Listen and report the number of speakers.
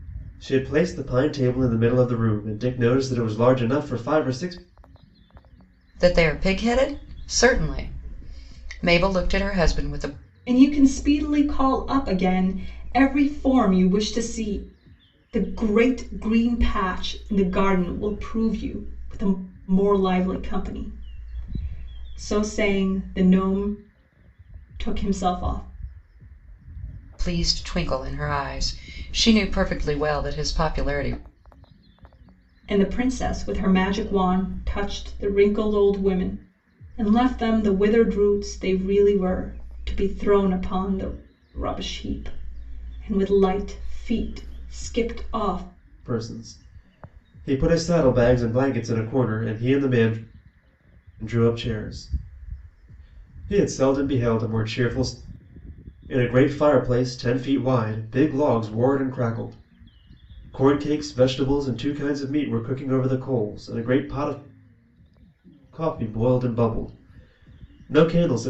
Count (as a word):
three